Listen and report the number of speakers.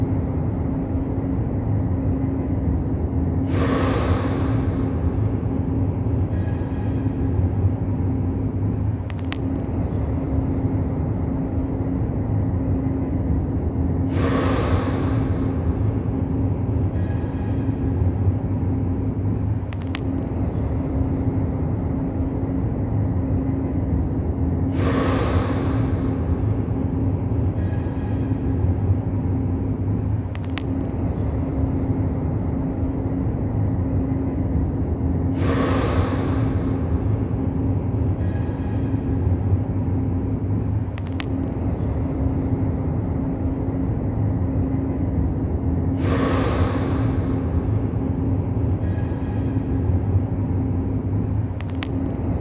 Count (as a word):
zero